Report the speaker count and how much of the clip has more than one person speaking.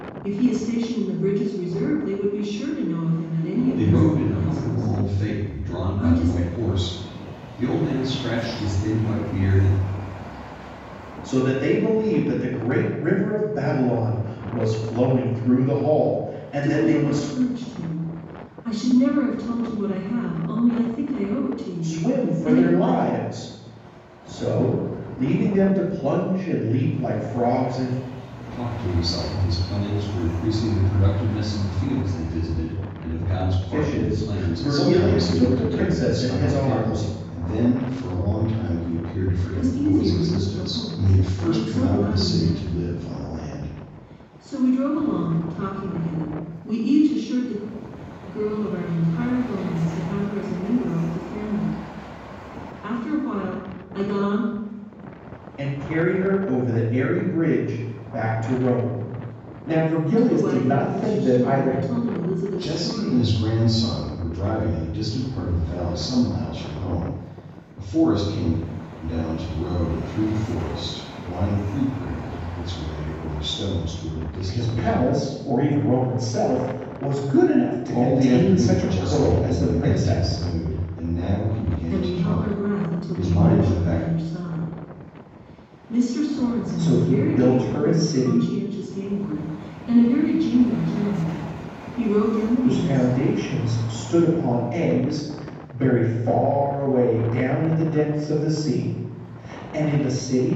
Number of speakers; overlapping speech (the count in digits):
3, about 22%